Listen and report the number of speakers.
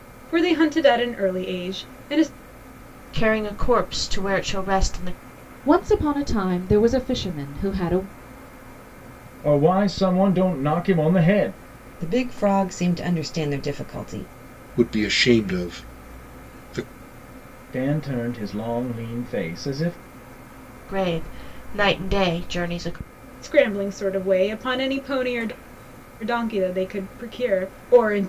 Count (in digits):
6